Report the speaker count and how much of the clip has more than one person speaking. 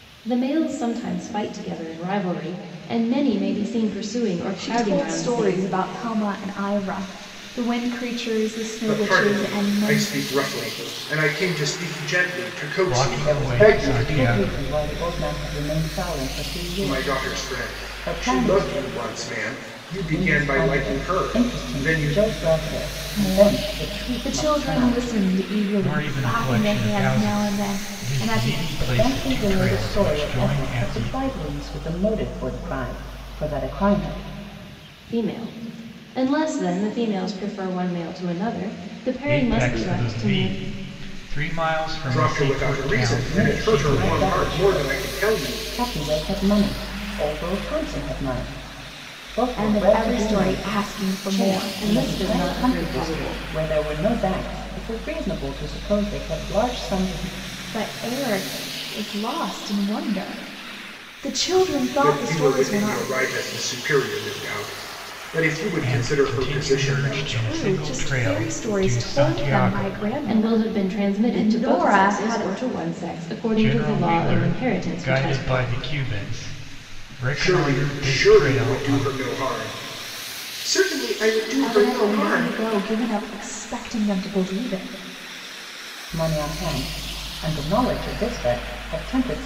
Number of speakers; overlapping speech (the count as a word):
five, about 40%